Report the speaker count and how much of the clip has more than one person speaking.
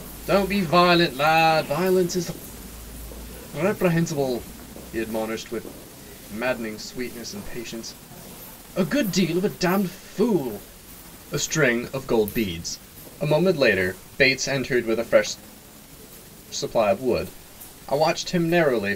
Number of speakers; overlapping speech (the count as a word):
one, no overlap